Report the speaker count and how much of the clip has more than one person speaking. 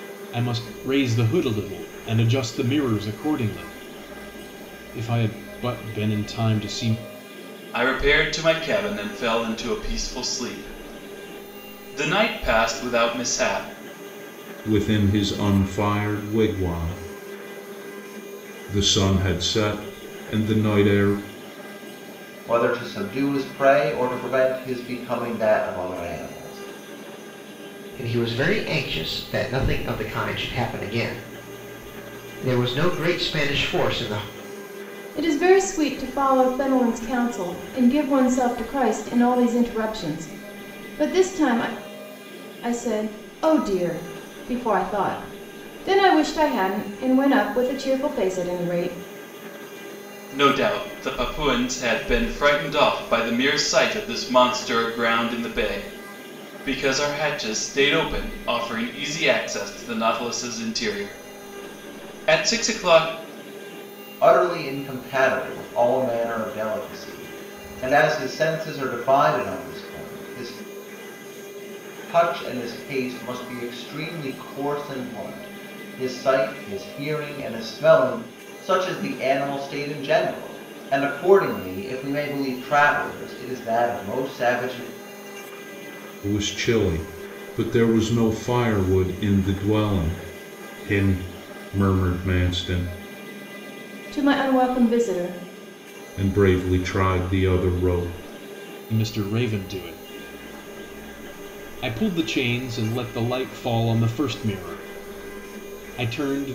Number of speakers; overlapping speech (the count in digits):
6, no overlap